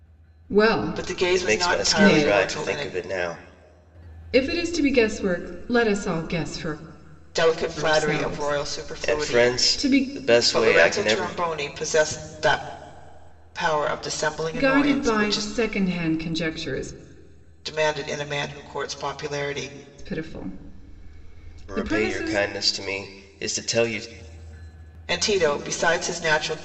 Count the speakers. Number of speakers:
three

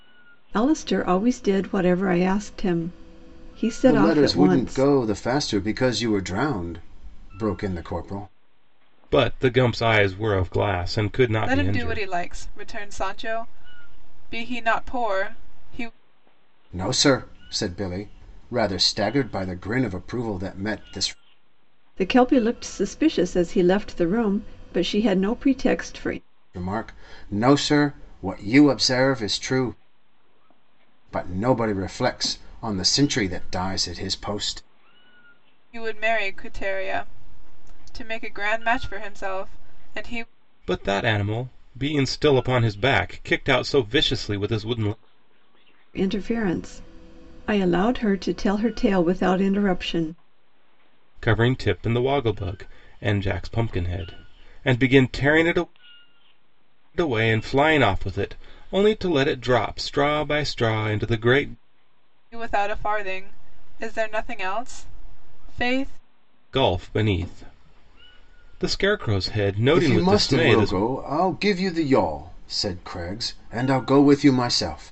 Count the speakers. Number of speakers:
four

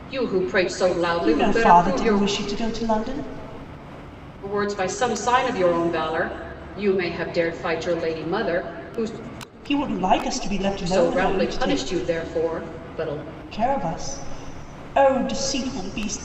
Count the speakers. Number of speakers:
two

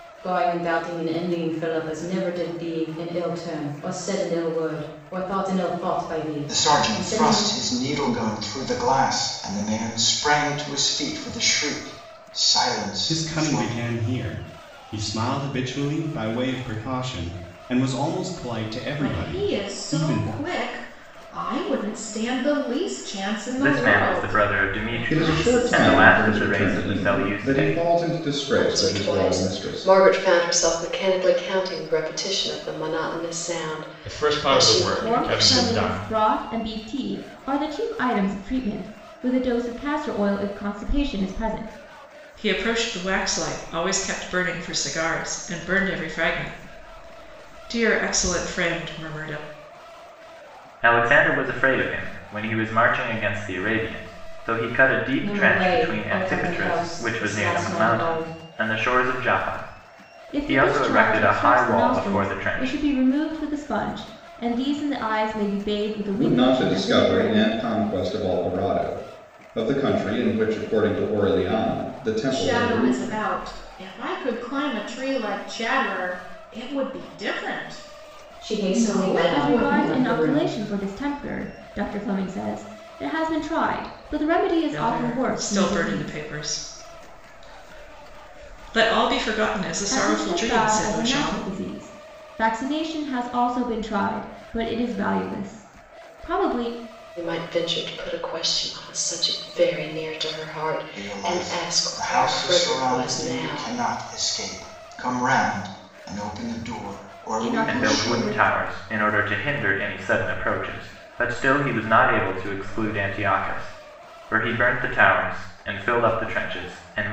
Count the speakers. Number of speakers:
ten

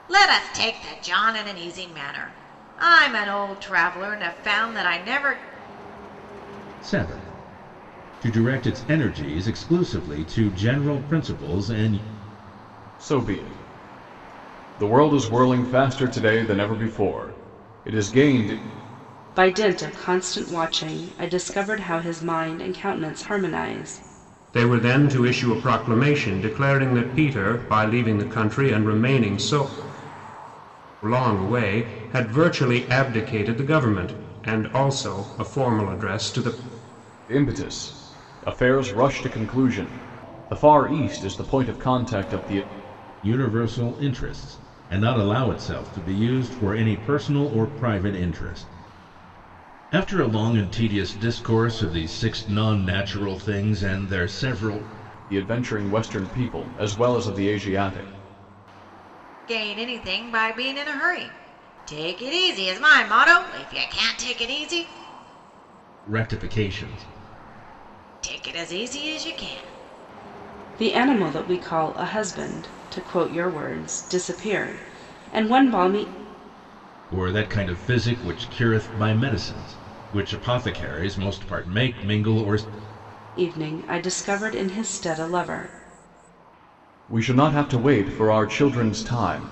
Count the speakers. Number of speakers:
five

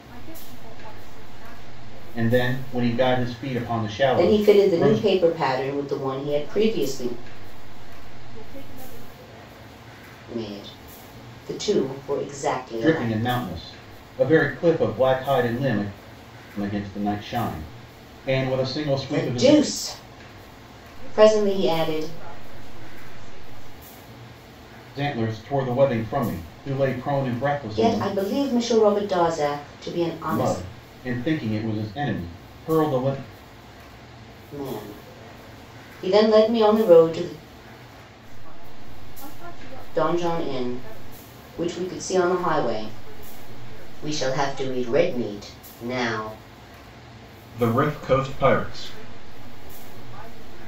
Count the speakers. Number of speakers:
three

